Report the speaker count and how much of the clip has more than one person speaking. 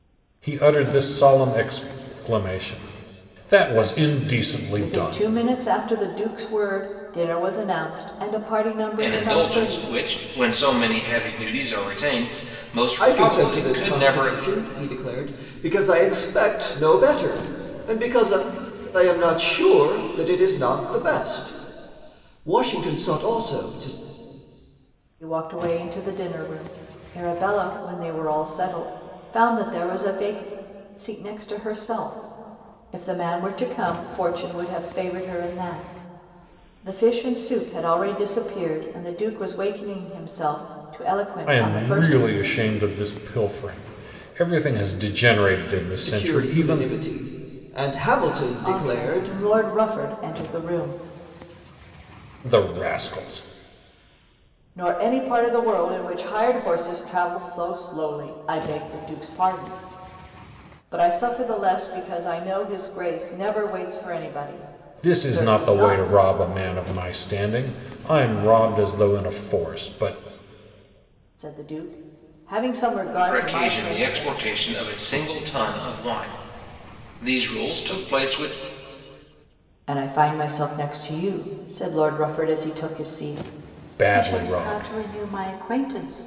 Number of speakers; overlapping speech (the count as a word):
four, about 10%